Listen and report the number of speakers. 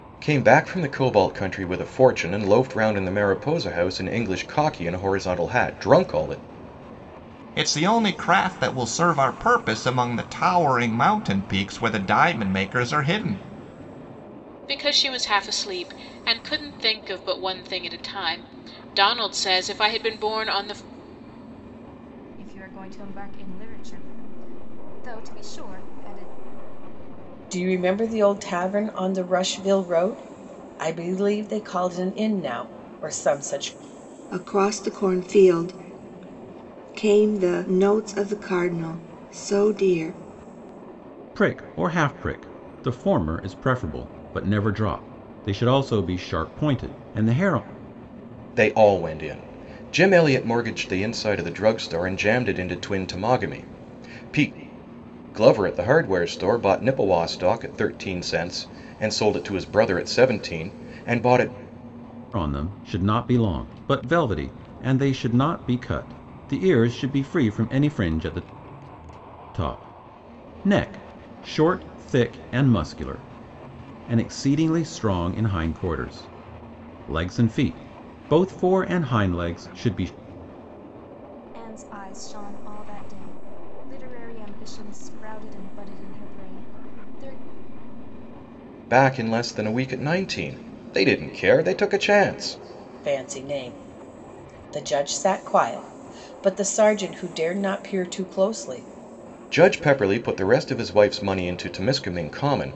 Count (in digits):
7